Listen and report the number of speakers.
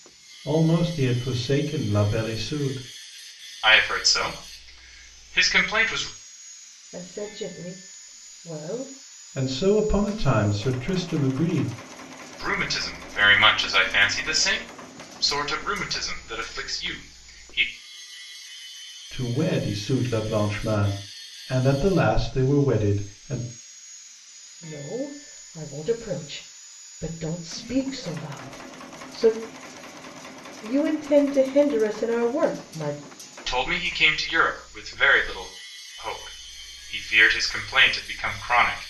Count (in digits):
3